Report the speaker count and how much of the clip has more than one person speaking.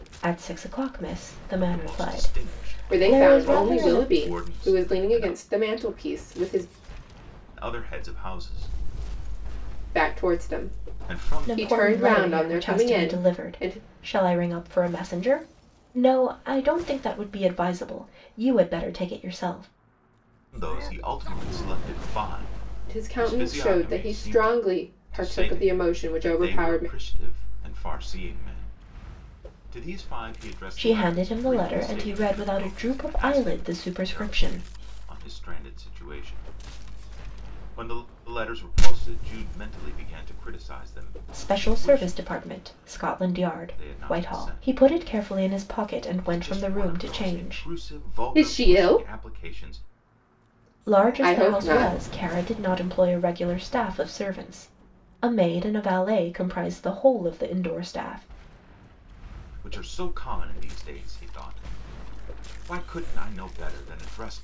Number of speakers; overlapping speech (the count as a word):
three, about 32%